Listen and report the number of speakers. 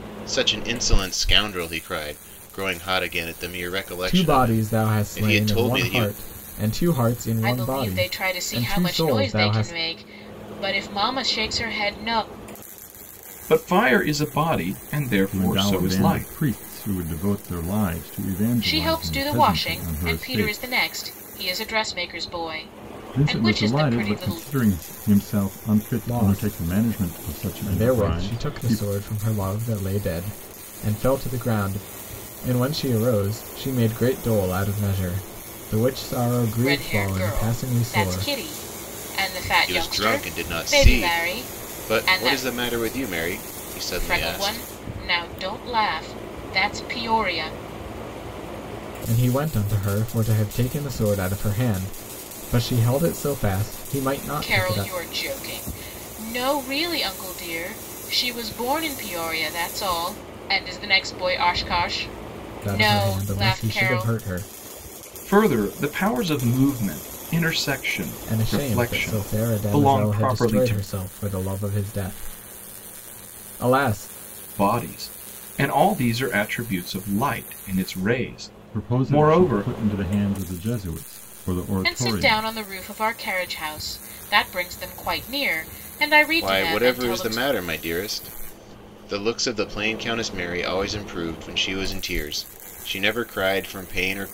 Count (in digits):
5